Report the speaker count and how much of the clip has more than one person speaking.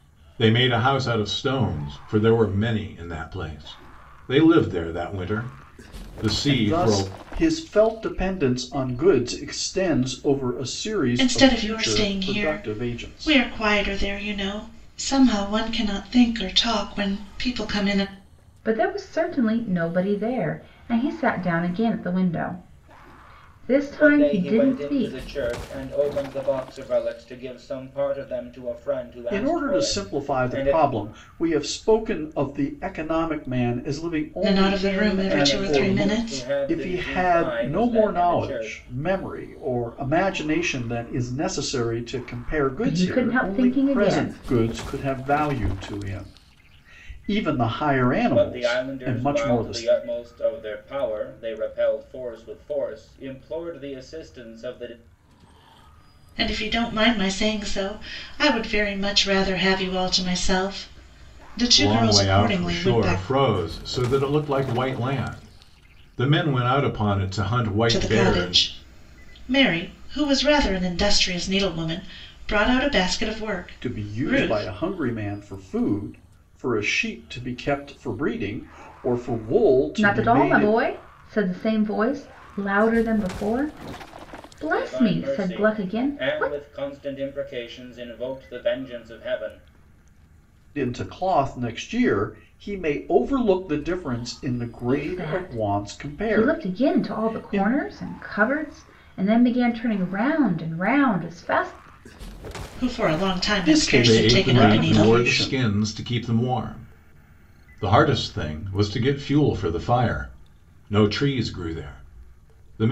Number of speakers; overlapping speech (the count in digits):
5, about 21%